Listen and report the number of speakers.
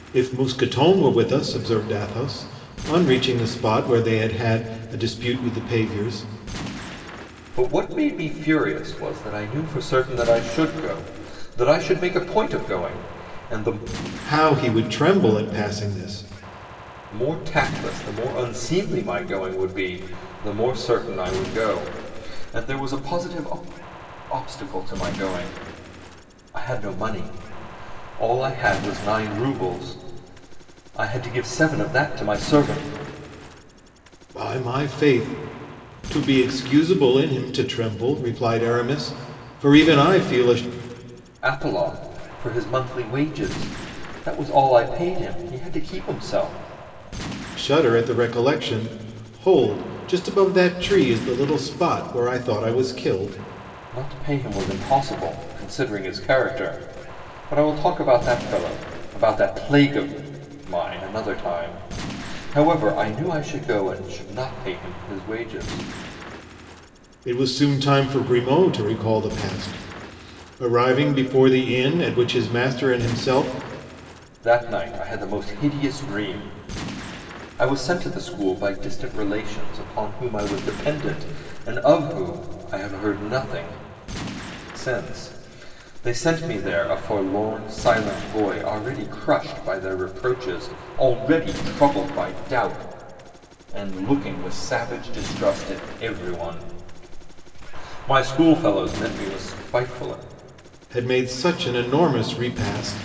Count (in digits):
2